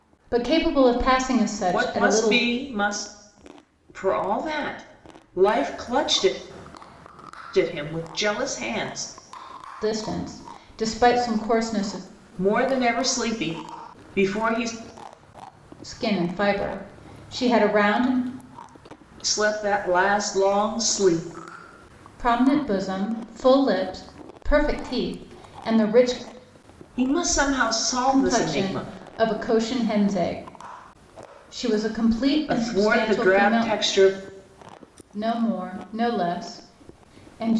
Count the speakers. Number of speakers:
two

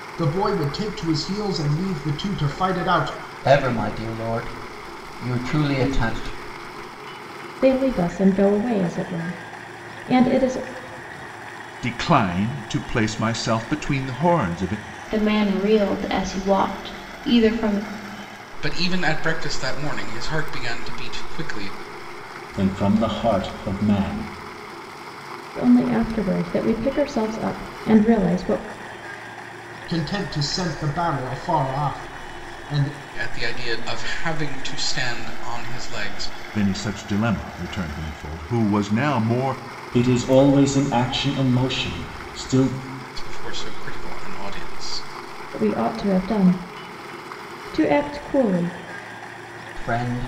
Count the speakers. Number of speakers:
seven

